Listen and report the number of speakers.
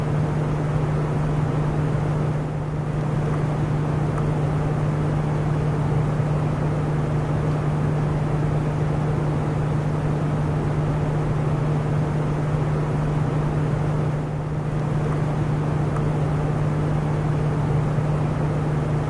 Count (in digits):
0